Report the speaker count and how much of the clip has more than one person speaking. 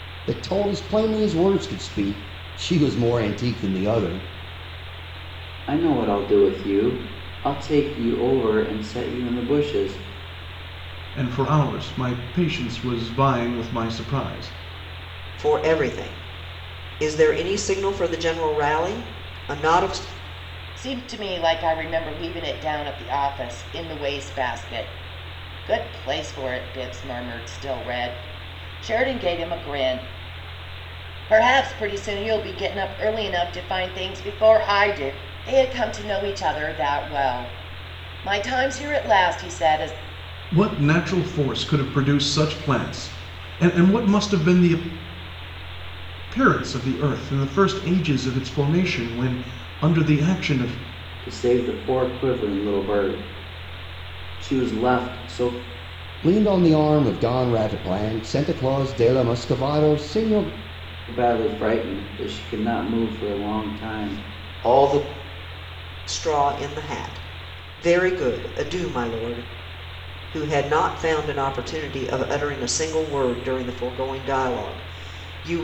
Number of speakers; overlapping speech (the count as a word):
five, no overlap